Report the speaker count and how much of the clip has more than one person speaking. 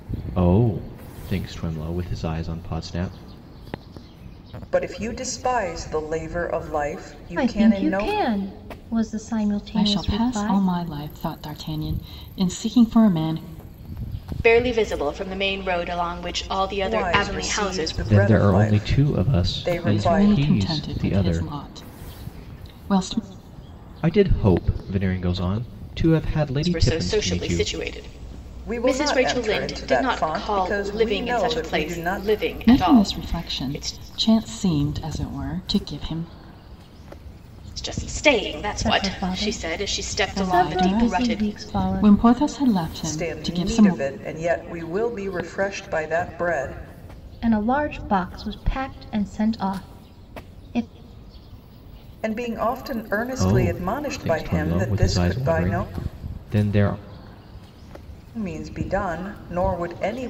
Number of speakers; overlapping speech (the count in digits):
5, about 32%